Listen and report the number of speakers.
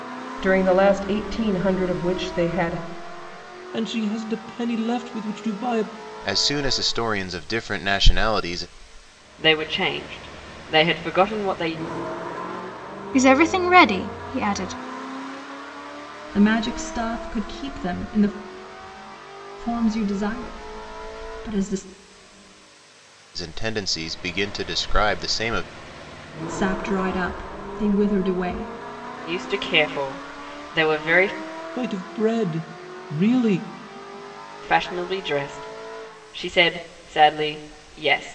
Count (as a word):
six